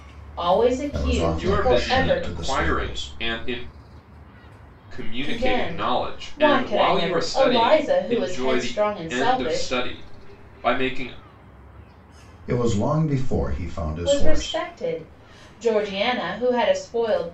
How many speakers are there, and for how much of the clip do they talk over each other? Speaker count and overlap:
3, about 42%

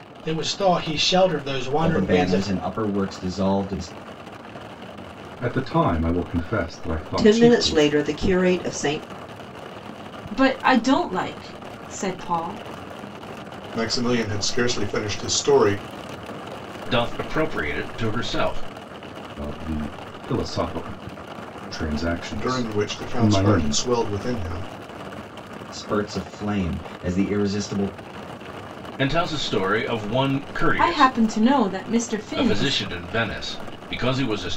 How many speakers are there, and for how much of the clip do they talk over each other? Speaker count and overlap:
7, about 11%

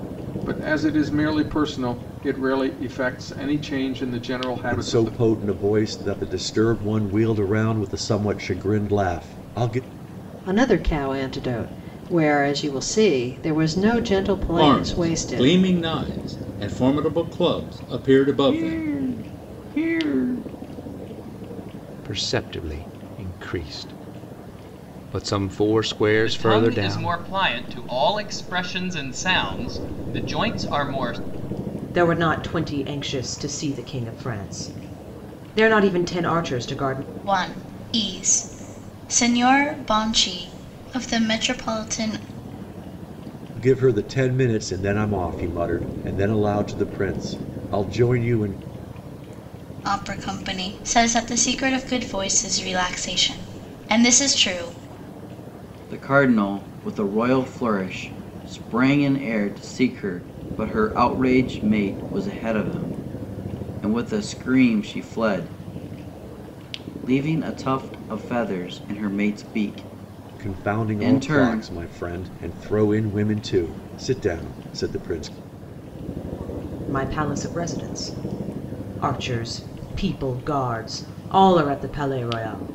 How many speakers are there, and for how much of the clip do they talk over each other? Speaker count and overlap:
9, about 5%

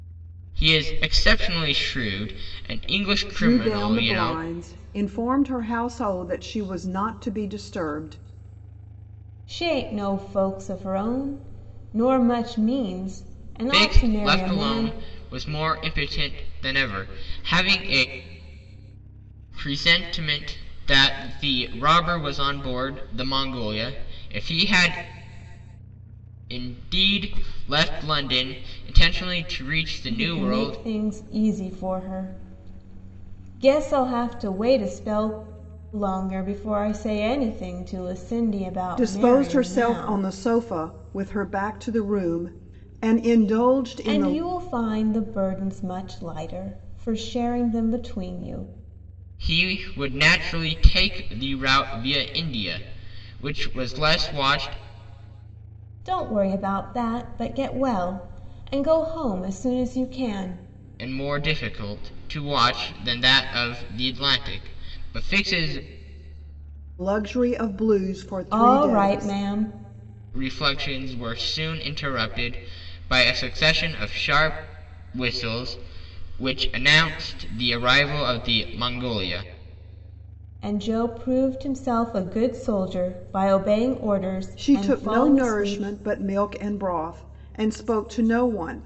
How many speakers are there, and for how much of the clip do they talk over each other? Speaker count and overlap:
3, about 8%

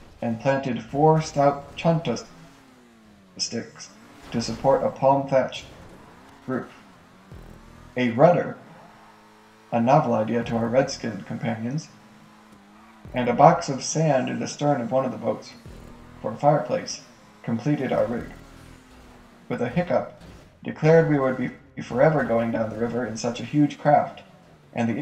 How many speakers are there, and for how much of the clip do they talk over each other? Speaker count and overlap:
1, no overlap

